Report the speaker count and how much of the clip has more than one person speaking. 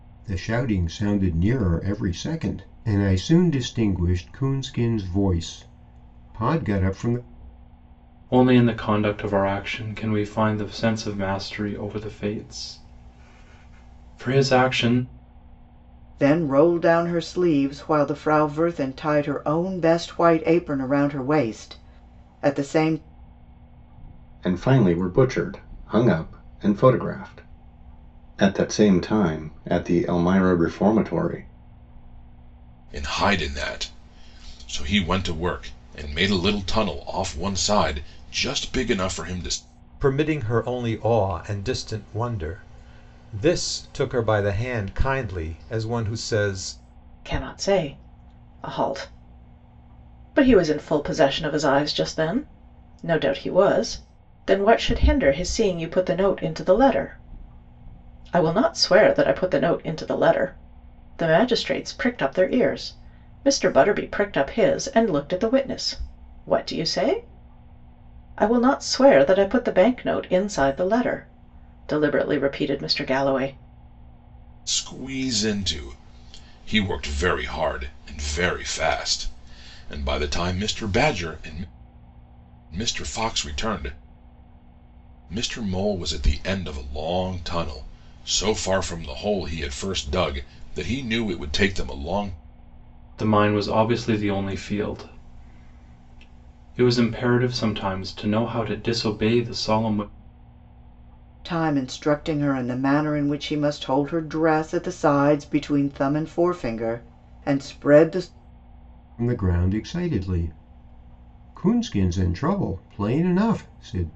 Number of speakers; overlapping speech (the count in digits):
7, no overlap